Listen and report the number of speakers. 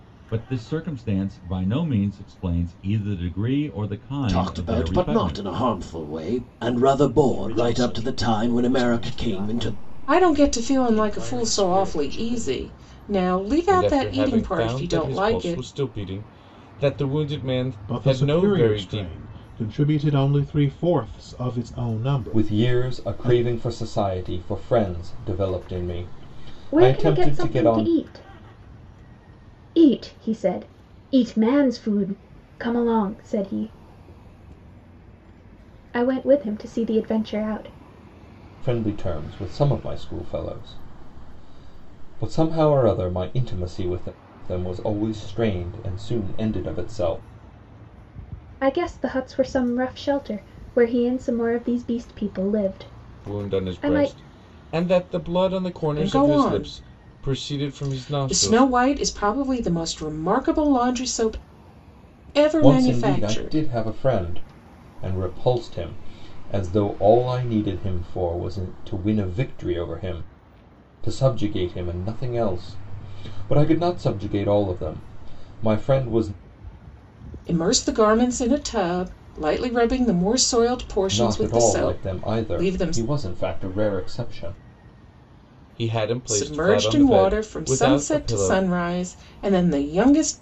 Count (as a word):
eight